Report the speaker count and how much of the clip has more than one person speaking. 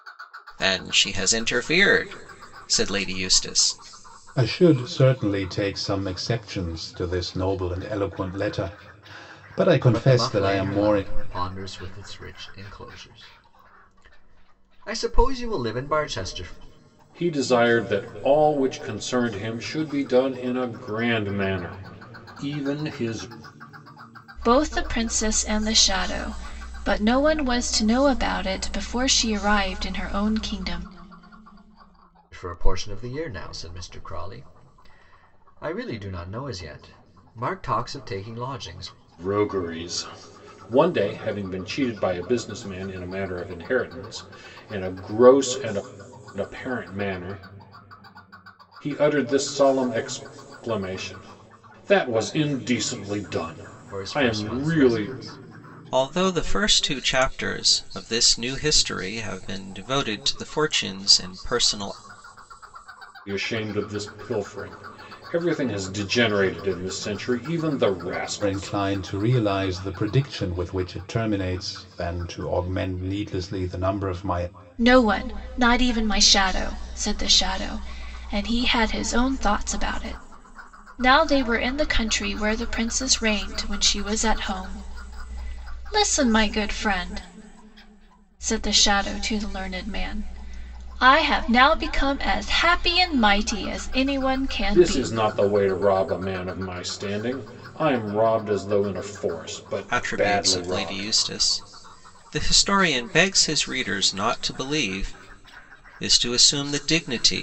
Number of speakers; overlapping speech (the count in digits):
5, about 4%